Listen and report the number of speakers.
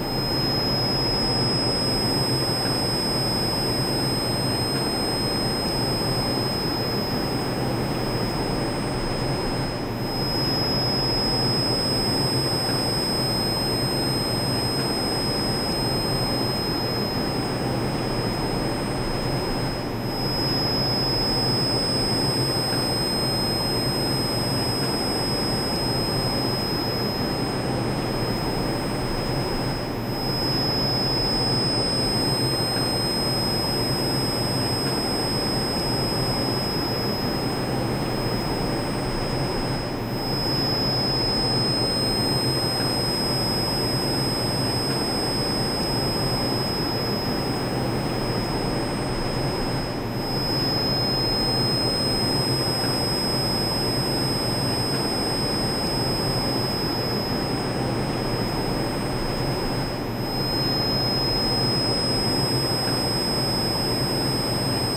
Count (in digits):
0